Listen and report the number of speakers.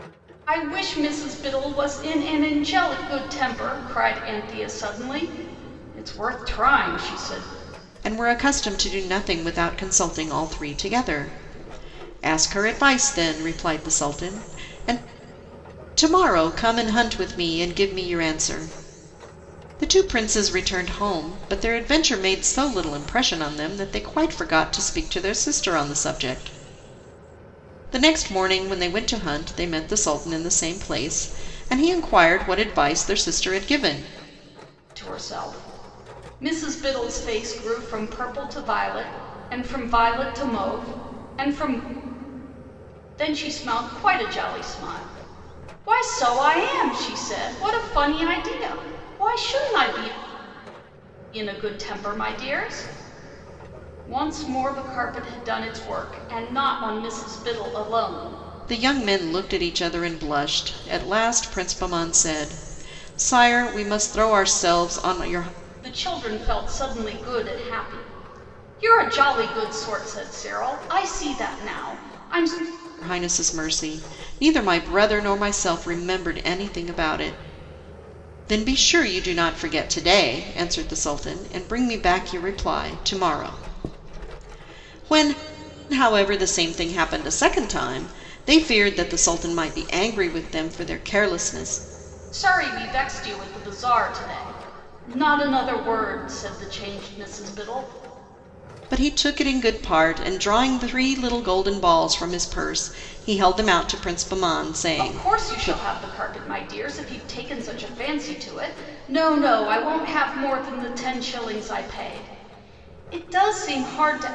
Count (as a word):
two